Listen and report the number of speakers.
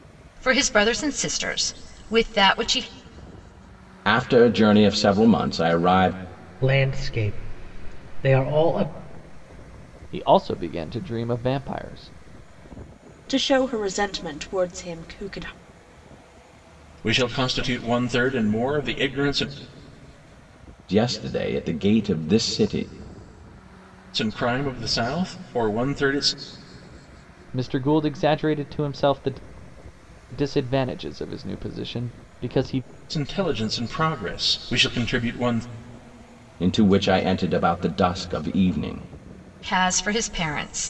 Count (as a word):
six